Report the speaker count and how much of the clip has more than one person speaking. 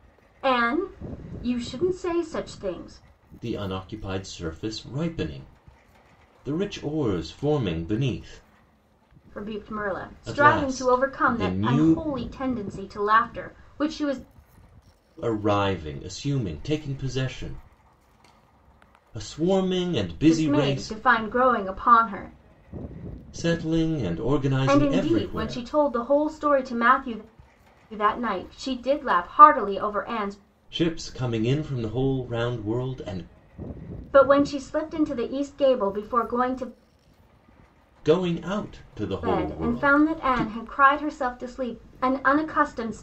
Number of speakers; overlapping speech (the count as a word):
two, about 12%